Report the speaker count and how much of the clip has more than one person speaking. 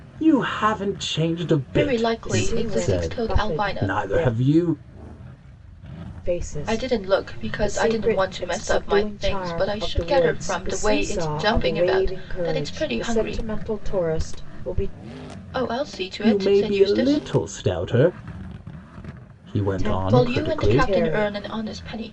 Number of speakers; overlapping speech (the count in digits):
3, about 55%